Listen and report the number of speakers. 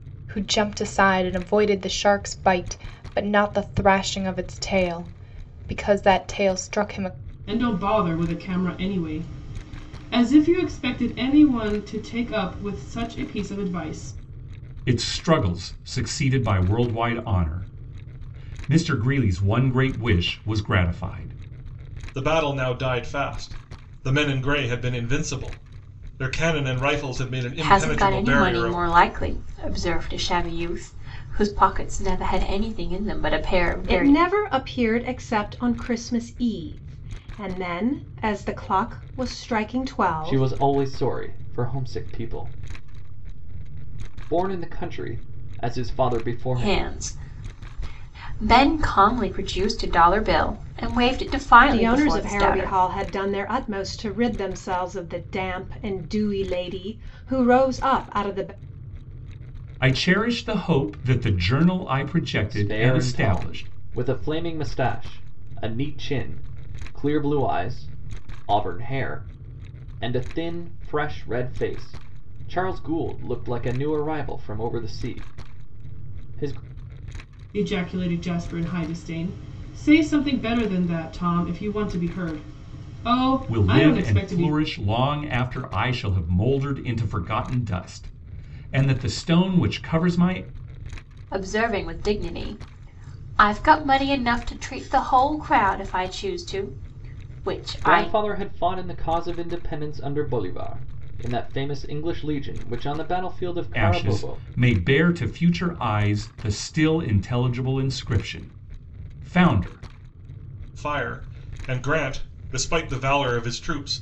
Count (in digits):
7